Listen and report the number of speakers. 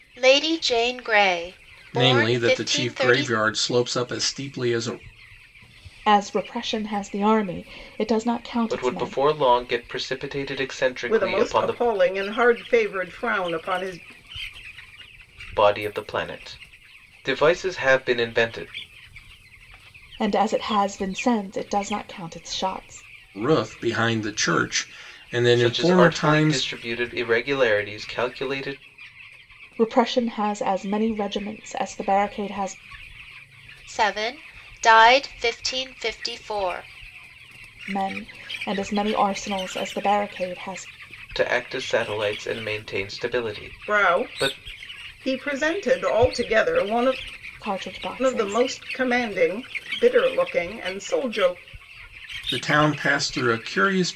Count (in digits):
5